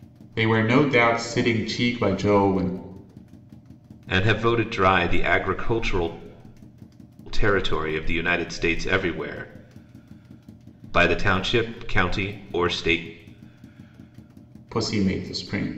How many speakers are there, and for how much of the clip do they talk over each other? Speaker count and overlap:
2, no overlap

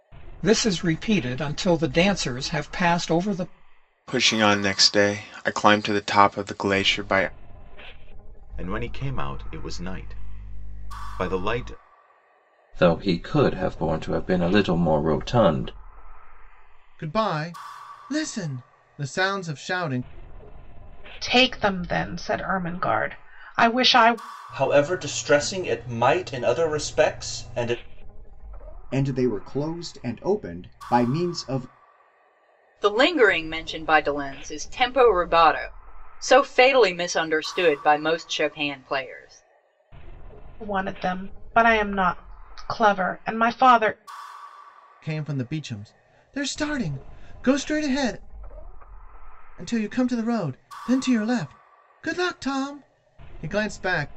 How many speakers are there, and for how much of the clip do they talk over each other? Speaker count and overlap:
9, no overlap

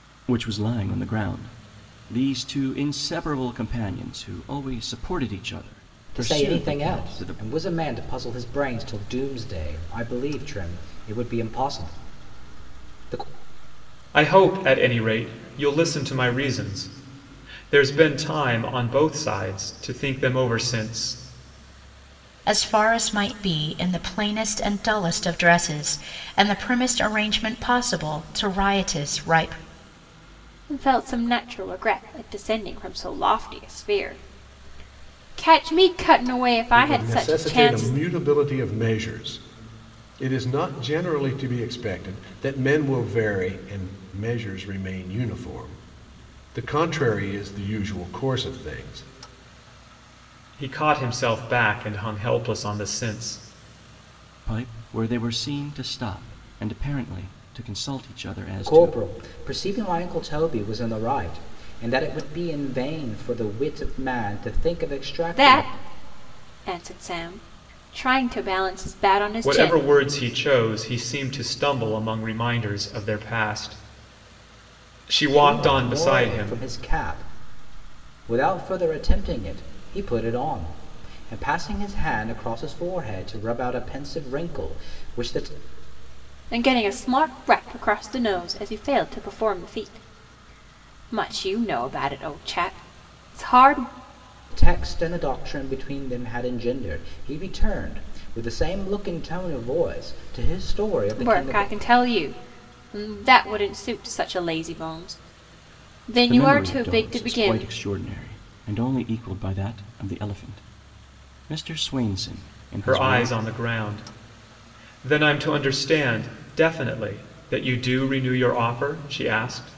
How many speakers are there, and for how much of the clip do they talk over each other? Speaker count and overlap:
6, about 7%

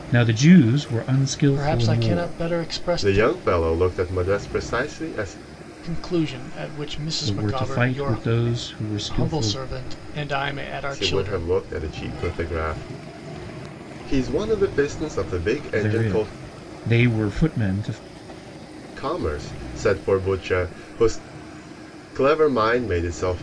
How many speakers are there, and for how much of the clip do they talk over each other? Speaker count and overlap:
3, about 17%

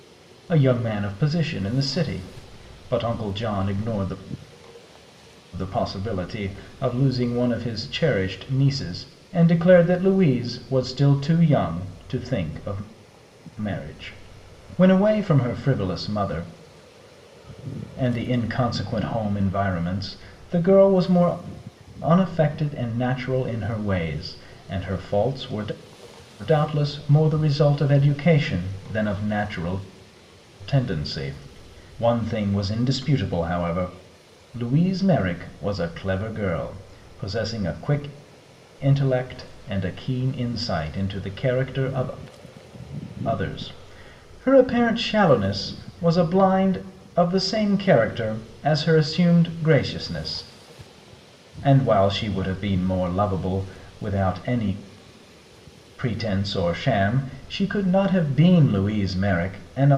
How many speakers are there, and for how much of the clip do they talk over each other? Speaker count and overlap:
1, no overlap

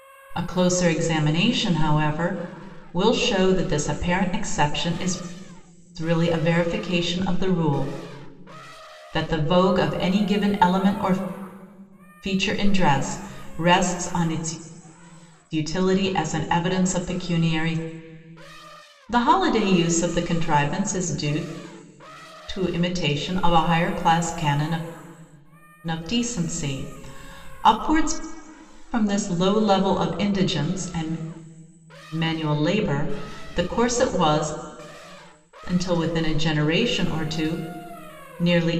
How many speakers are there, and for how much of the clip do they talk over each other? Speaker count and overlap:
1, no overlap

